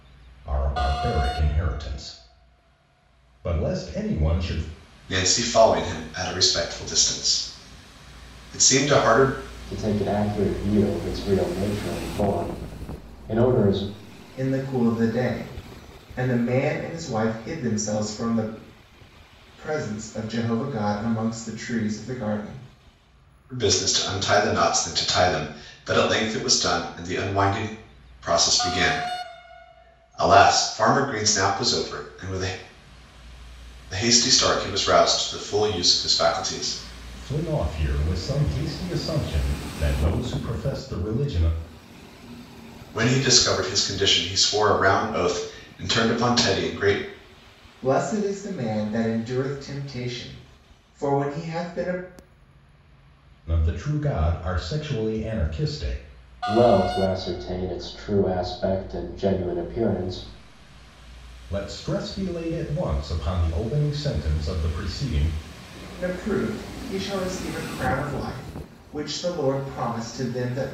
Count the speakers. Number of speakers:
4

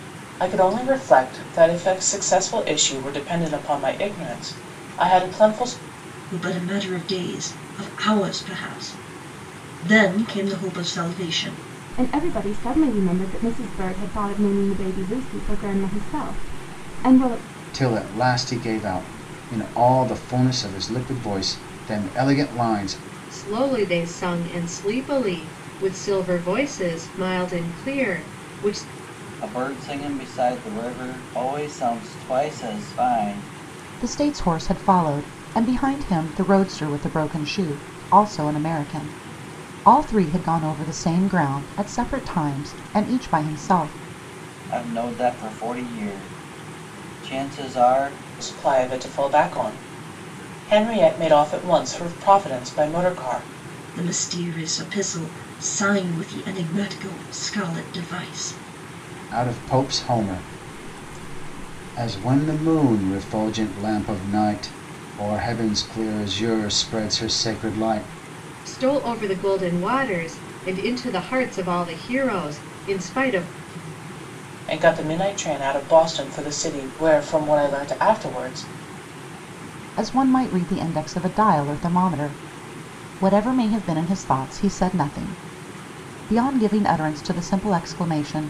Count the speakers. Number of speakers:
7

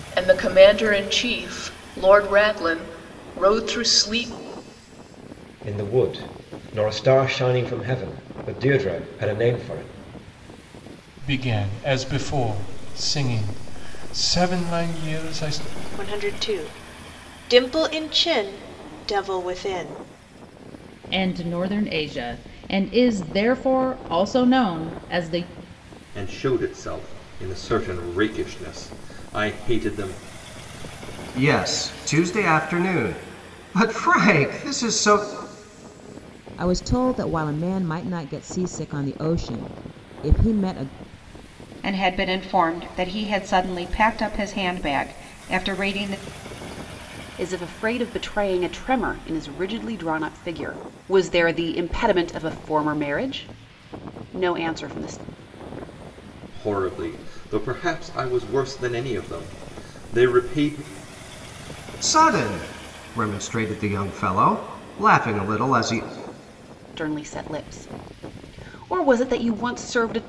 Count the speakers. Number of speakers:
10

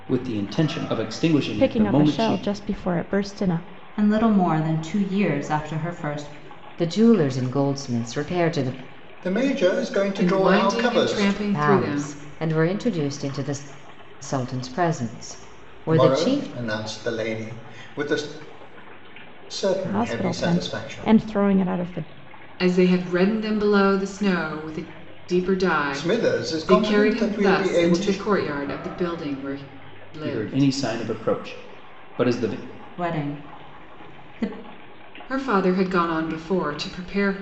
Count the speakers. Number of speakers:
6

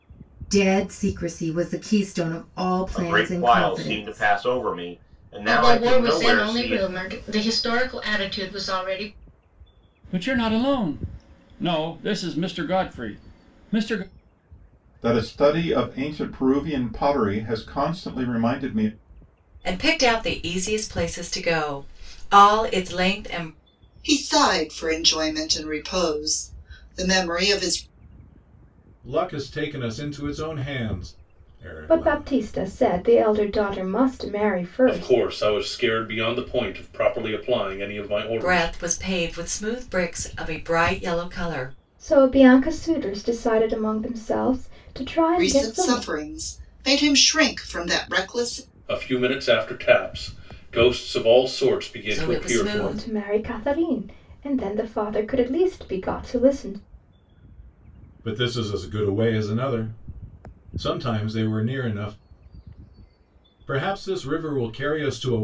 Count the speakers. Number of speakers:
10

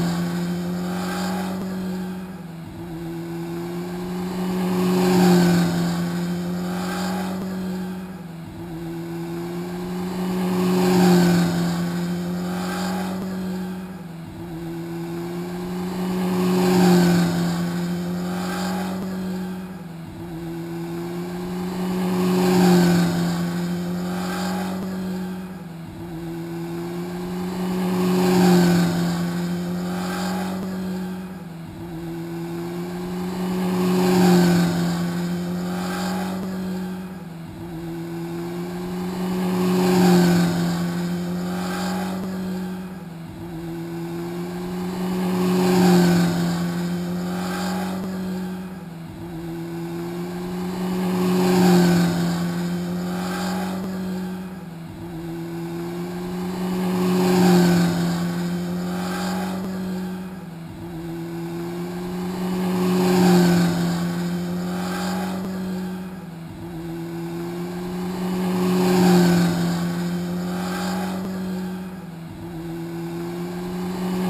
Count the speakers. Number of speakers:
0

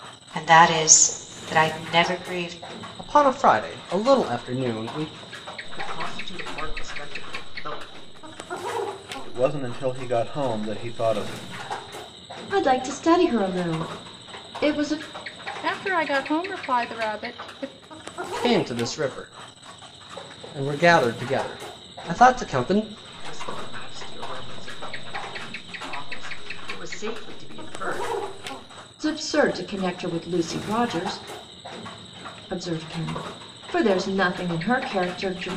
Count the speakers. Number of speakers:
6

